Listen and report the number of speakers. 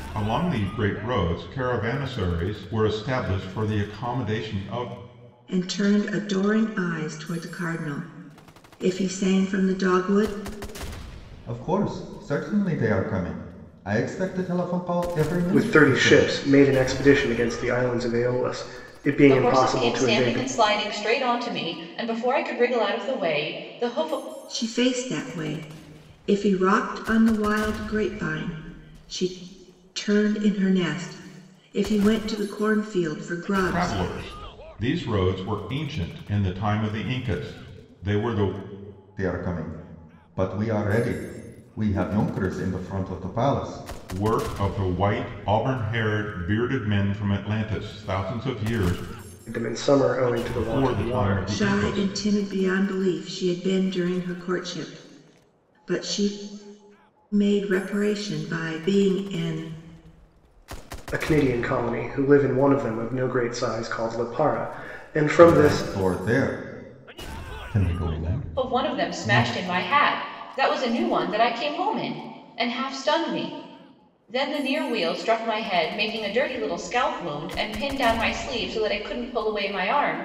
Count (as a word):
five